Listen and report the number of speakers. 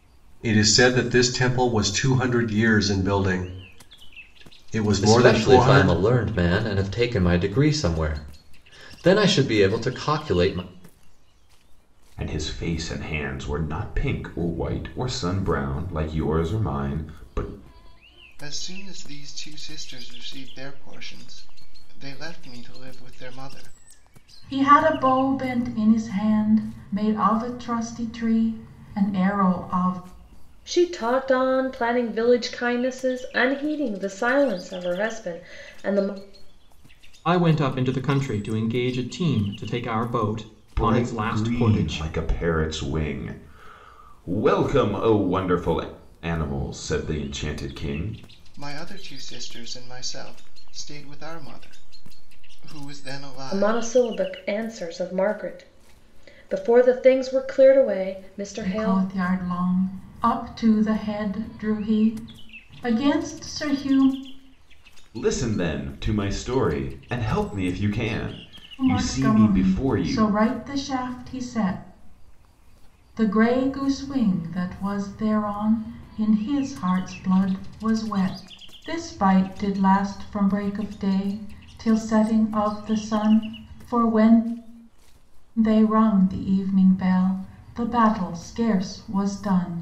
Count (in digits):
7